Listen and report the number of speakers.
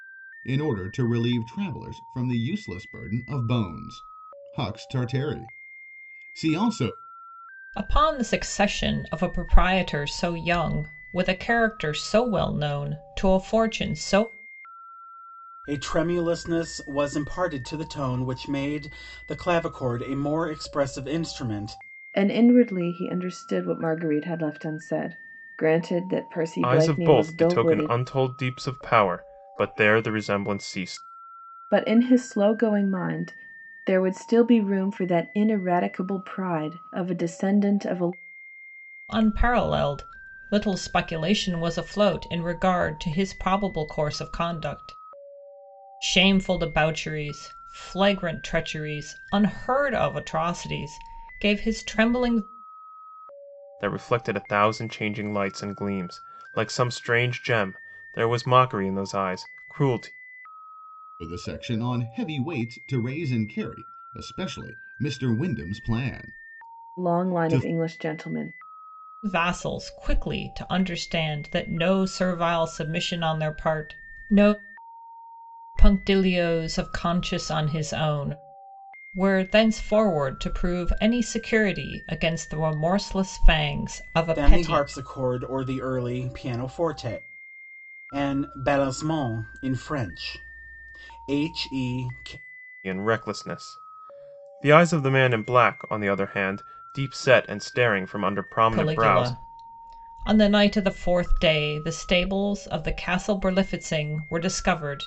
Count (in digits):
5